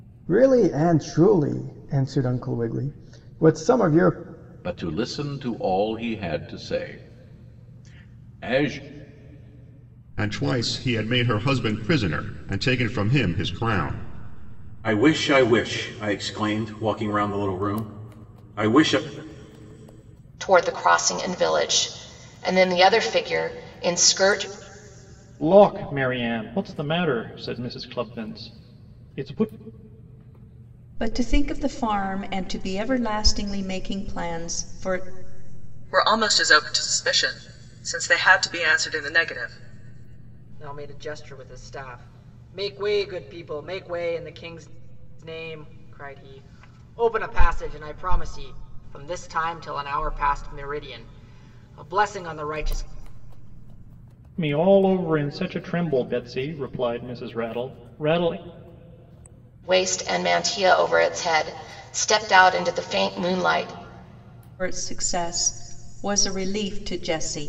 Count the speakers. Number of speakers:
nine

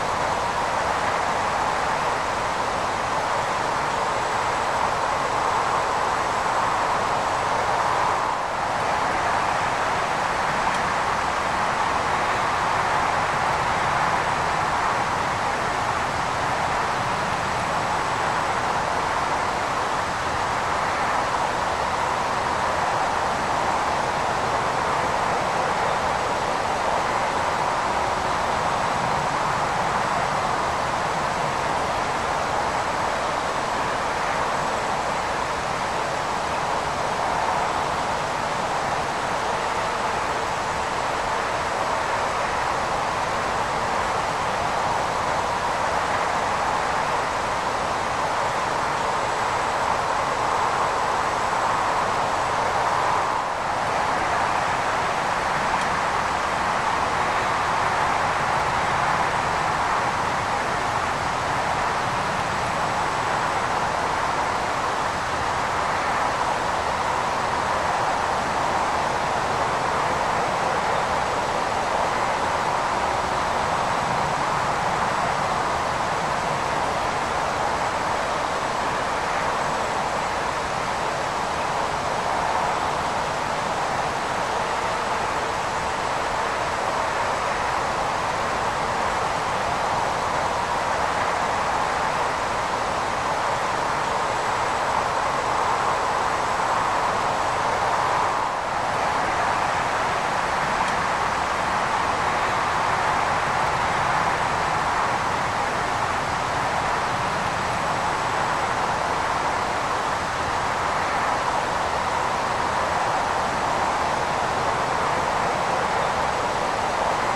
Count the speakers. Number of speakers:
zero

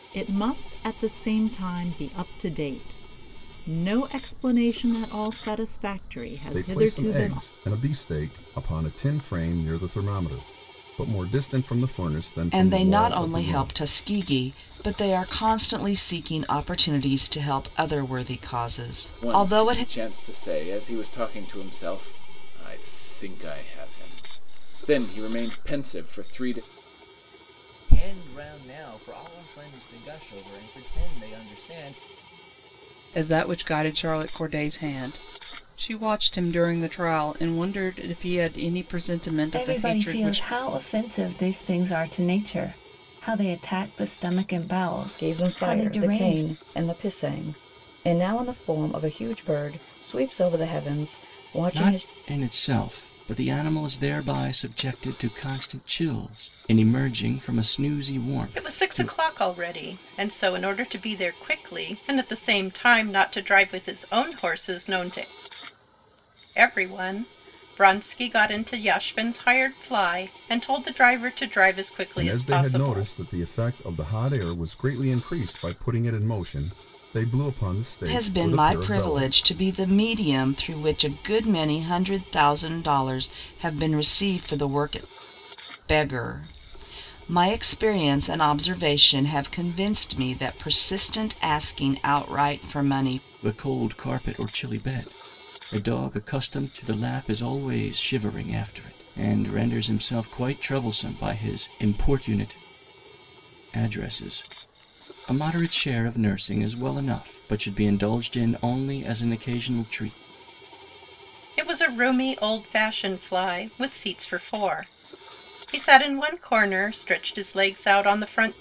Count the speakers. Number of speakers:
ten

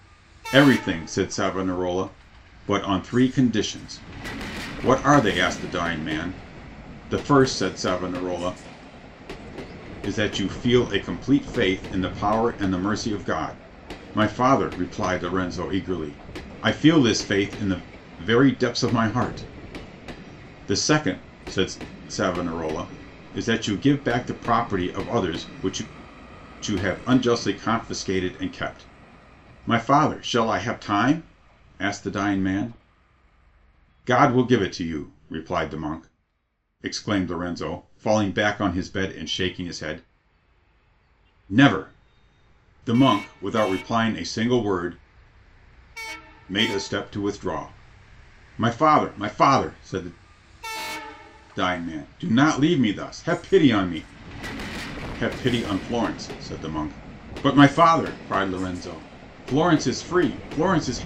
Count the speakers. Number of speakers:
one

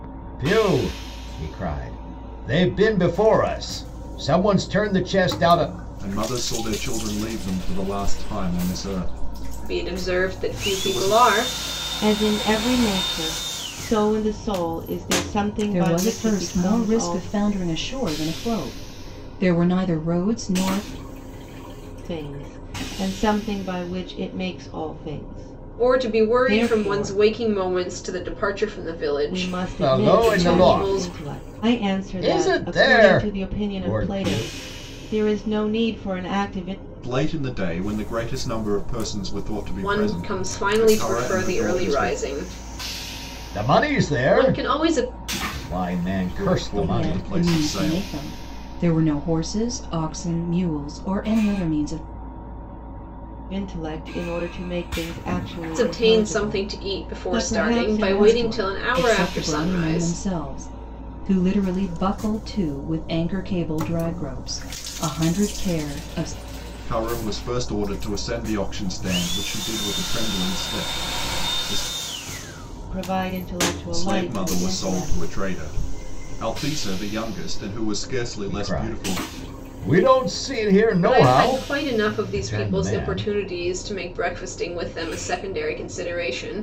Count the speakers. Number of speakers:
five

